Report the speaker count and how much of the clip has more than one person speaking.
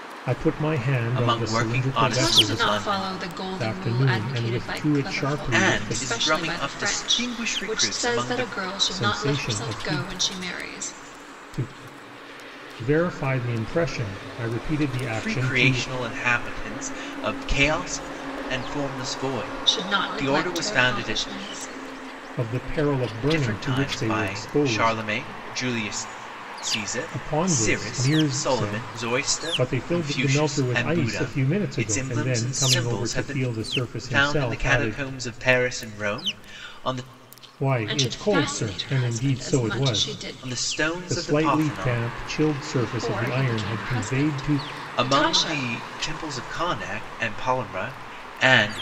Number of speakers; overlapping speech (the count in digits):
3, about 56%